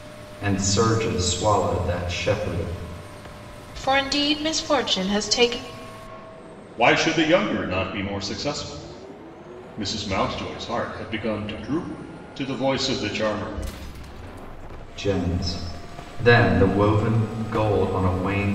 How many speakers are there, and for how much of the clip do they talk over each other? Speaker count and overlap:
three, no overlap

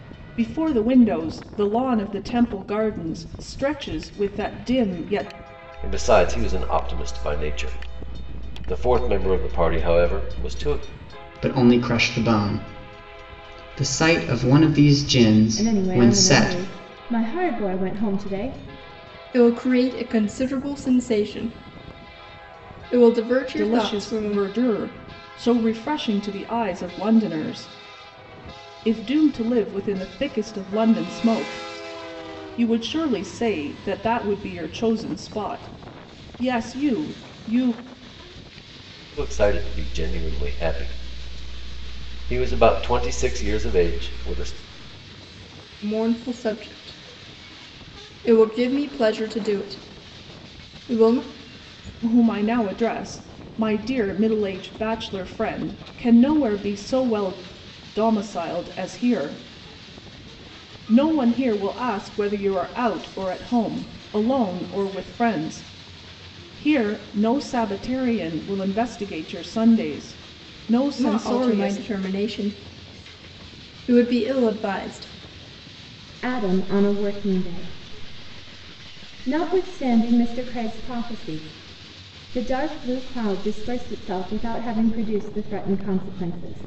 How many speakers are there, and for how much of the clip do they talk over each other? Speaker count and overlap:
five, about 3%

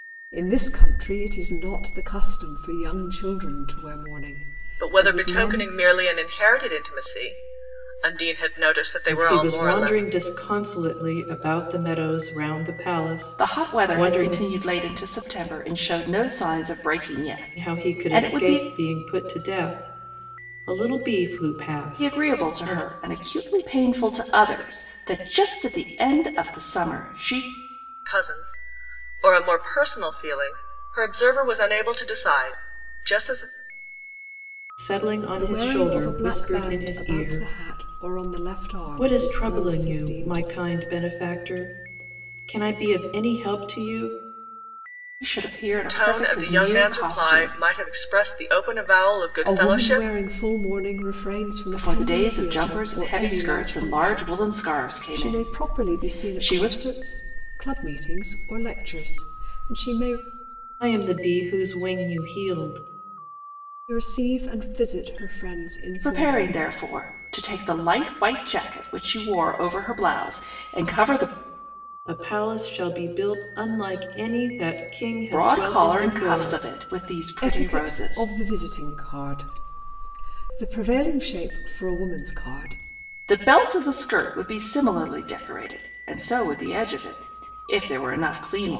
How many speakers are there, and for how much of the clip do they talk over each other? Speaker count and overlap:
four, about 21%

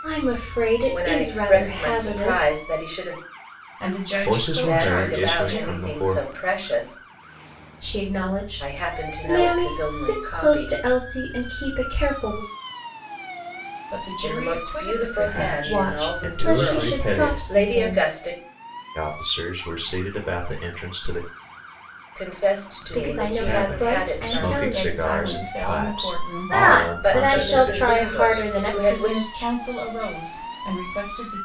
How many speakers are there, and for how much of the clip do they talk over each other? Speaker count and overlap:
four, about 52%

